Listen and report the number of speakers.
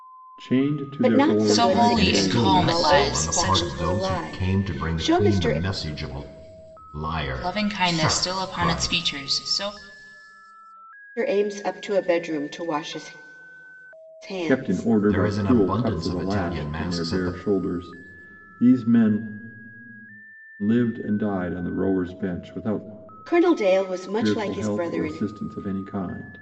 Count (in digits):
4